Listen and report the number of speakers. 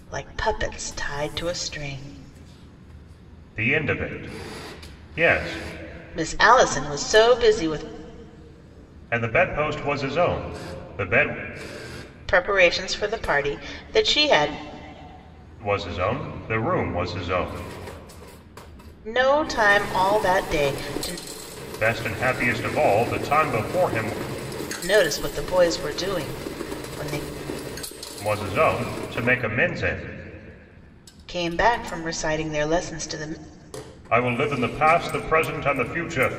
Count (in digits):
2